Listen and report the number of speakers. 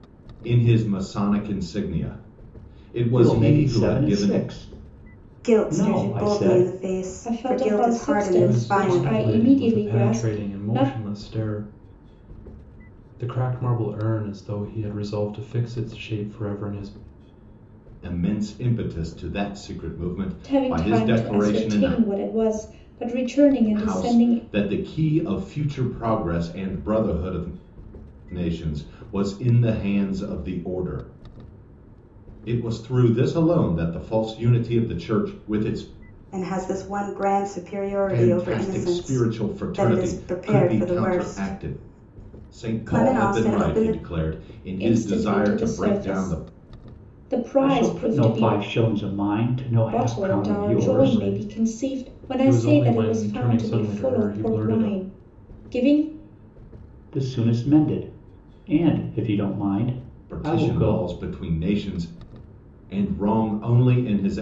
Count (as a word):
five